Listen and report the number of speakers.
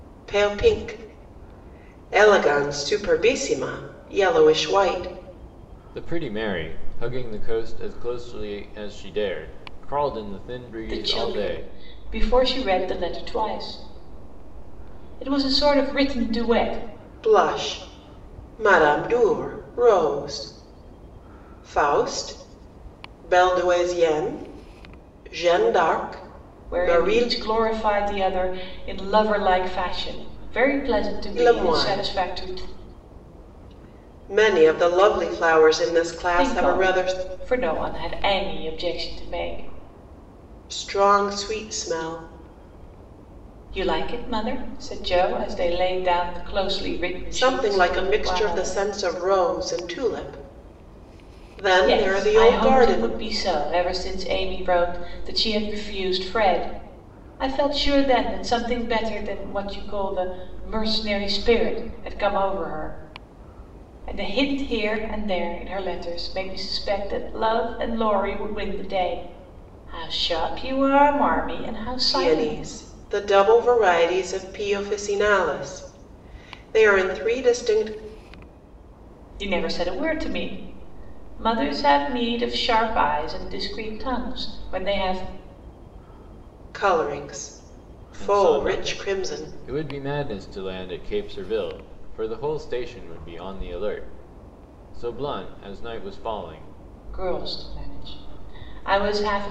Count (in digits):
3